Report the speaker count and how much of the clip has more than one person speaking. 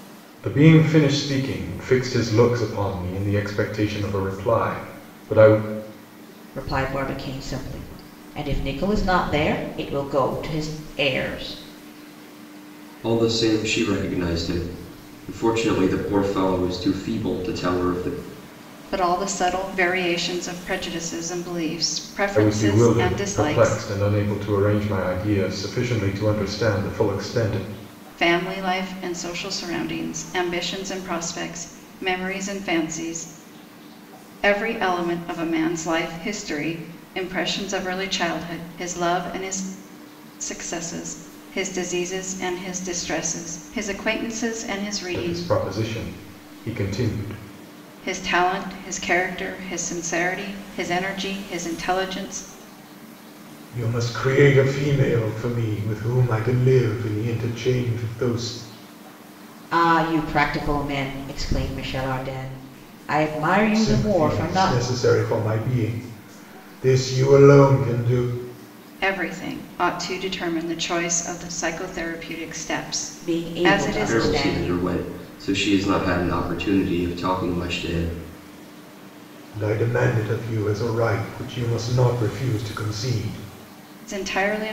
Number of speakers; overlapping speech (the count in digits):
4, about 5%